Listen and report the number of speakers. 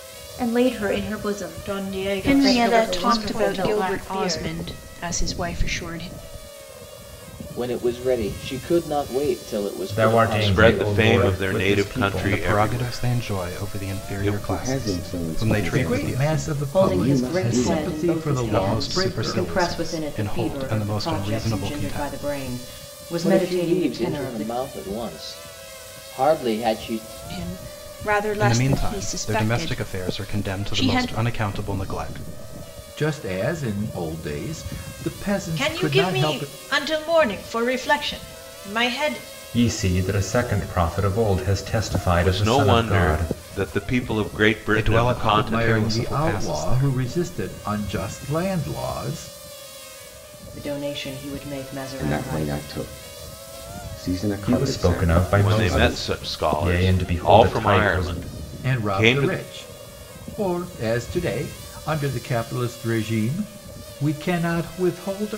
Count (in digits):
10